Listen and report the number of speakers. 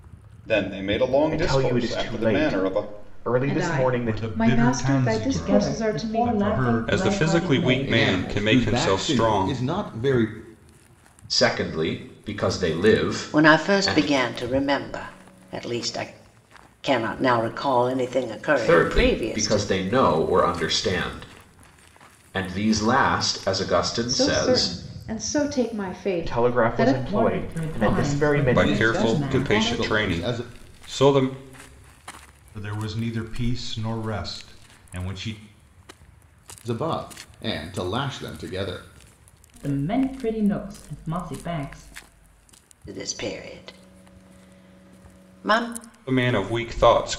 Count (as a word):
nine